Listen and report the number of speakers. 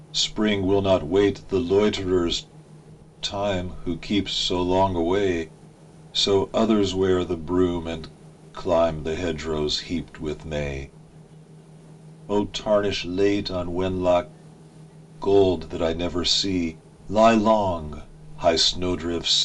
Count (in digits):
1